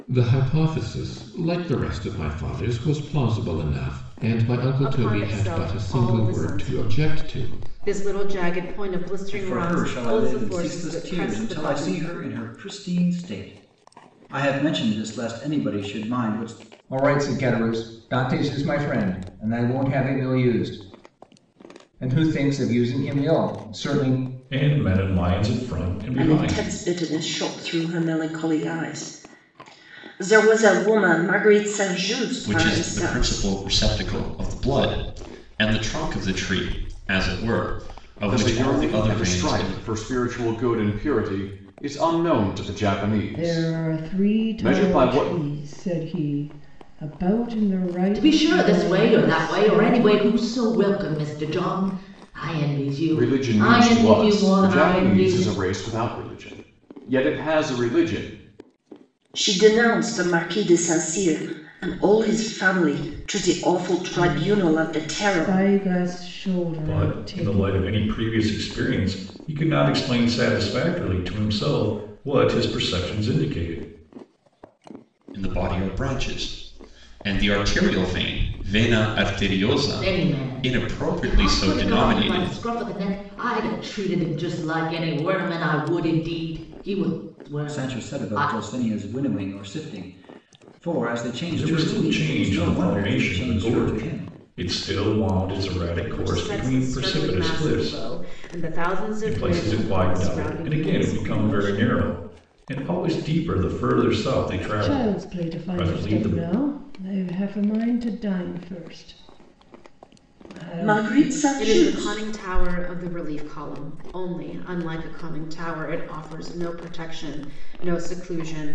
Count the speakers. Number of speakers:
ten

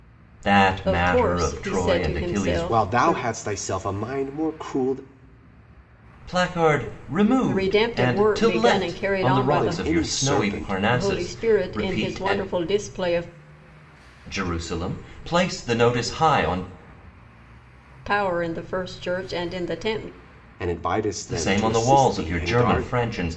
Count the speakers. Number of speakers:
three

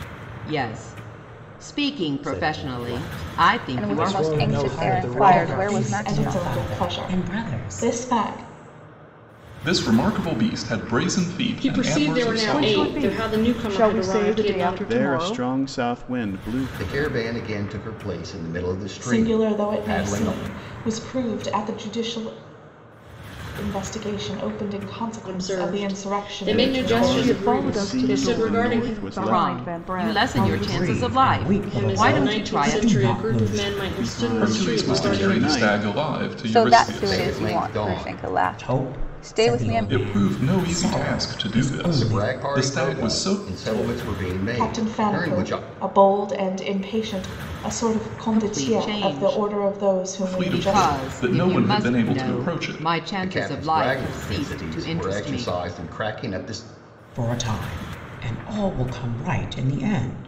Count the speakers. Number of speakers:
ten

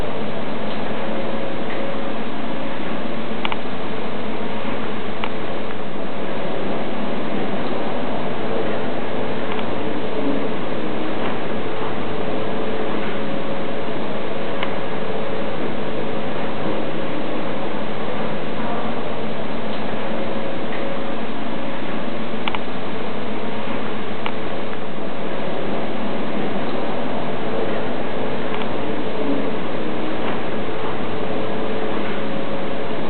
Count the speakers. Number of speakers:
zero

